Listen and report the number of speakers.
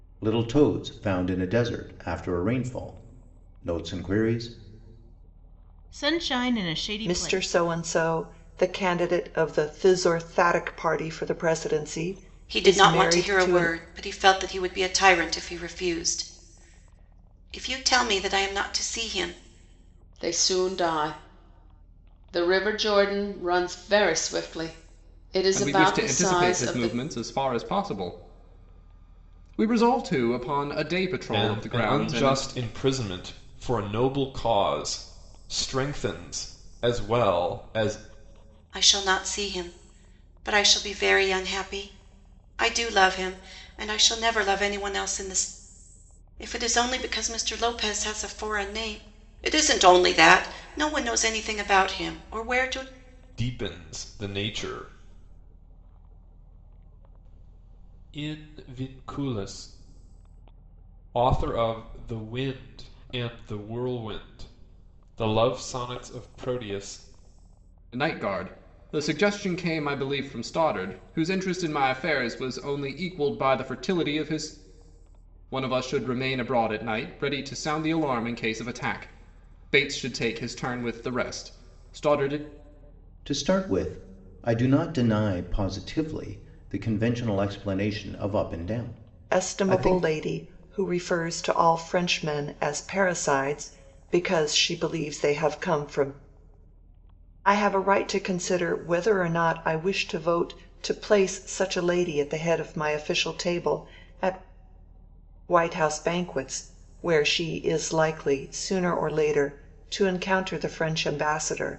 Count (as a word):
seven